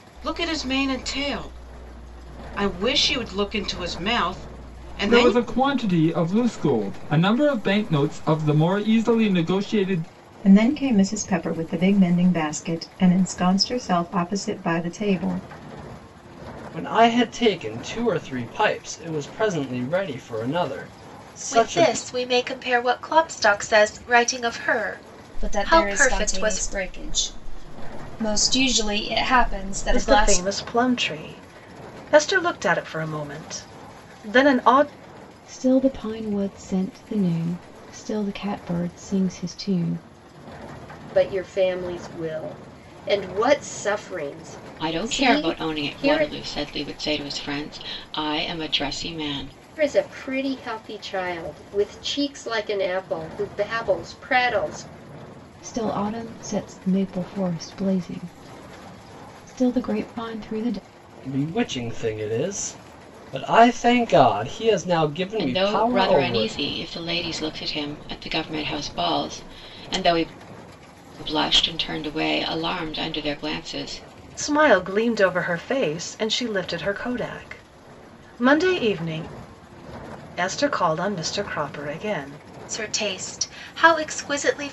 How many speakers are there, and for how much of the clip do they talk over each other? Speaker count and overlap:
10, about 6%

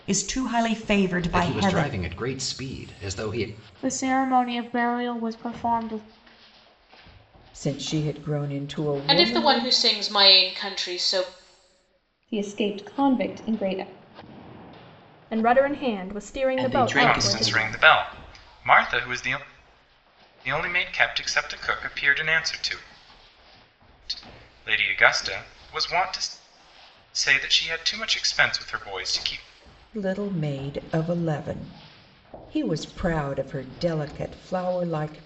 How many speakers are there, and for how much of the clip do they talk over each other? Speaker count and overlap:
9, about 8%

